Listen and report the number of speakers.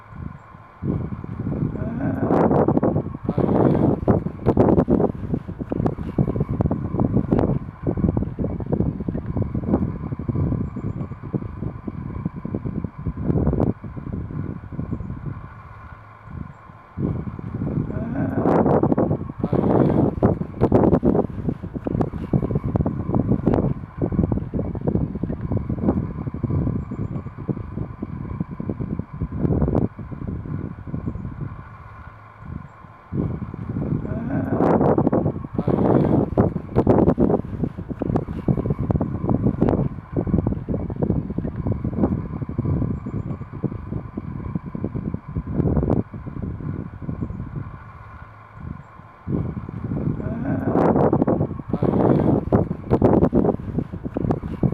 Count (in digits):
0